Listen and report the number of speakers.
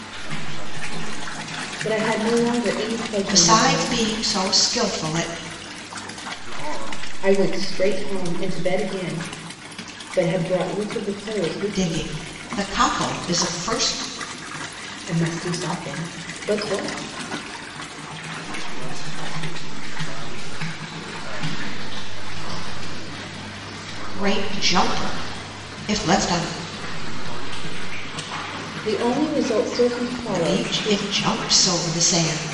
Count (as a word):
three